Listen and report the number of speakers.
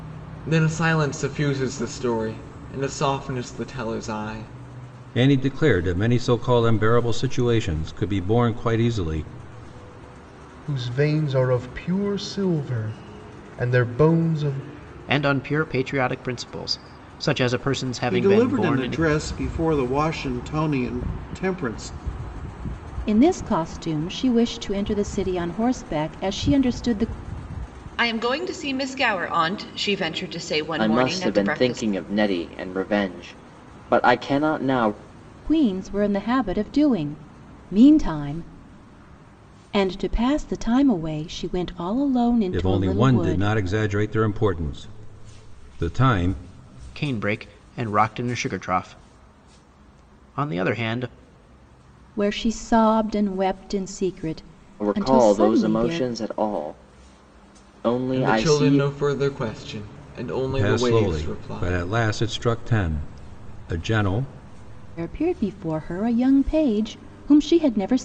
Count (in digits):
8